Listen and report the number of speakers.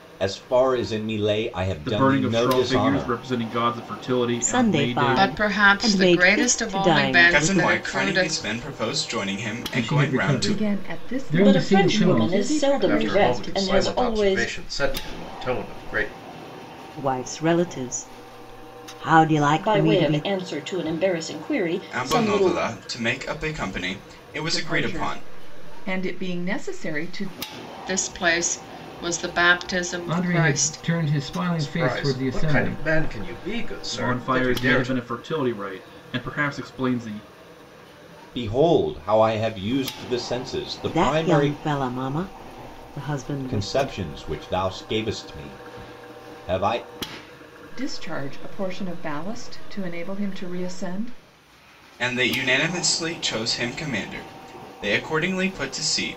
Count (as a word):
nine